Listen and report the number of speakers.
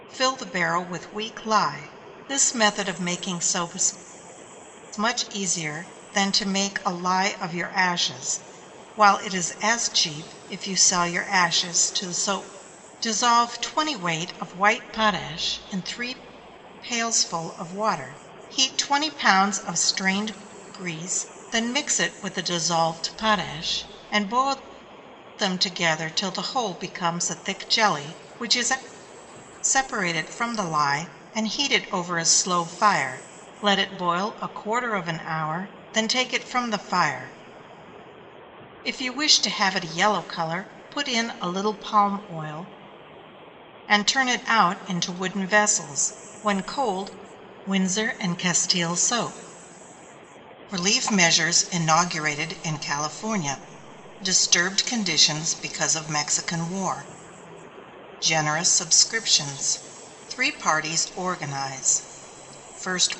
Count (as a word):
one